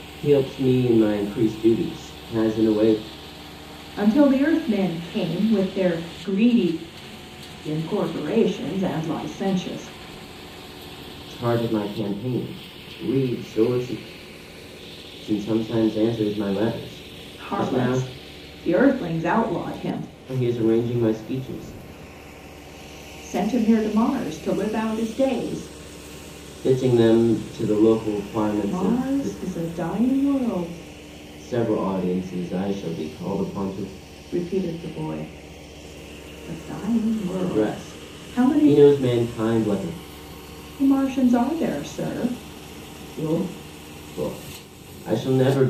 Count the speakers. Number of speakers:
2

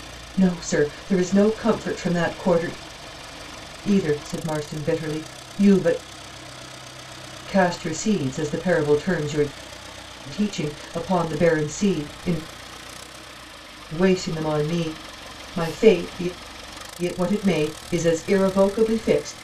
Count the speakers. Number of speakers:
1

